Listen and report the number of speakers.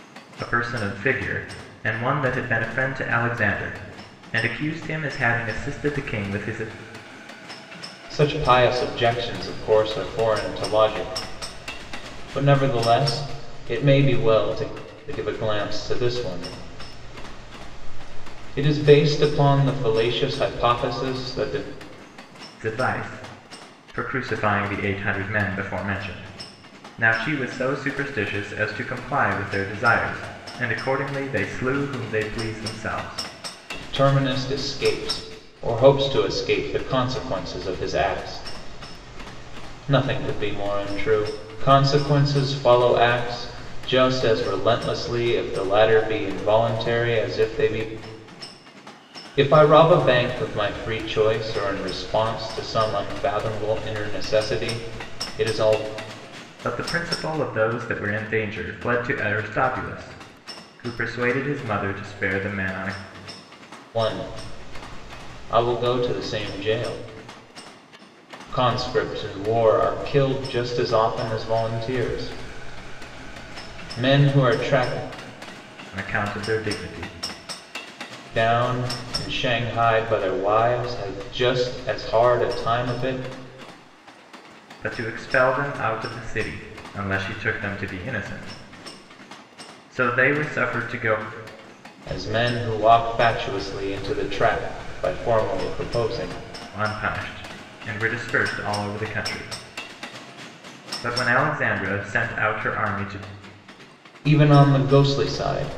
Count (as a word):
two